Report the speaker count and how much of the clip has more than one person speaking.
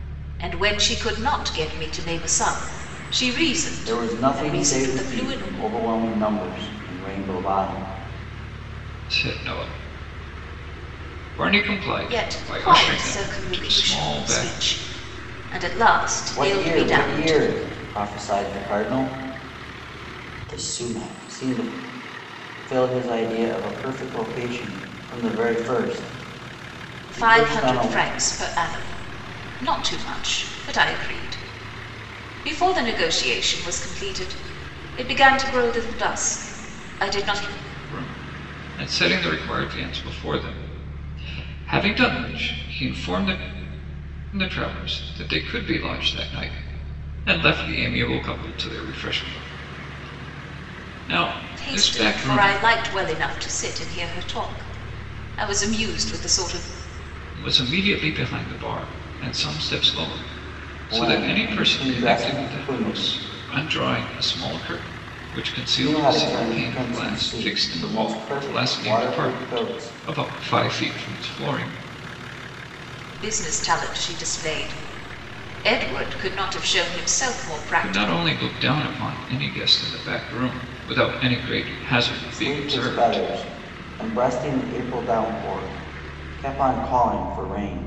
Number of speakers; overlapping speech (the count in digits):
3, about 18%